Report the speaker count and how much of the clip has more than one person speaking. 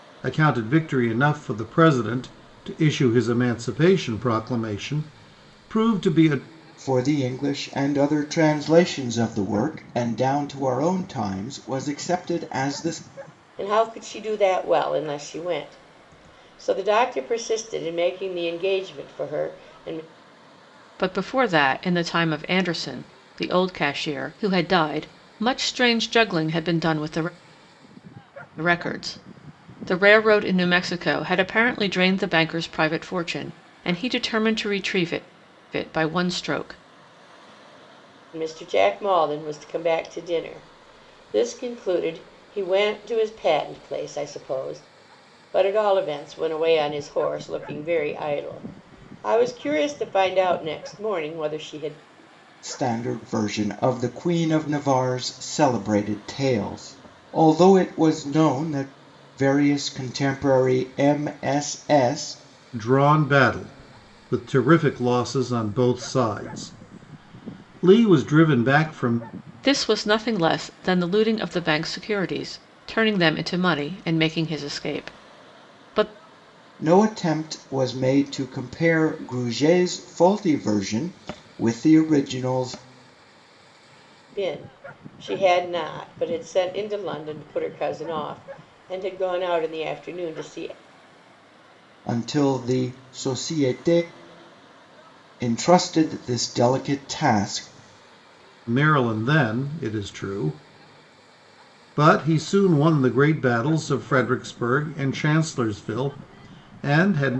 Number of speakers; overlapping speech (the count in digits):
4, no overlap